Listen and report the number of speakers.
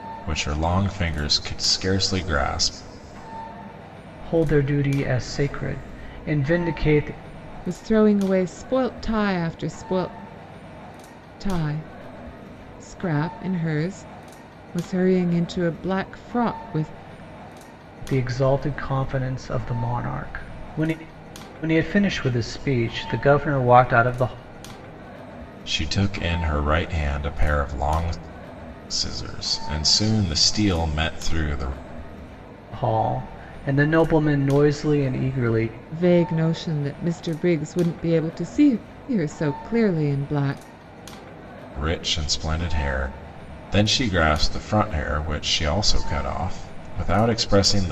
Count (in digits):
3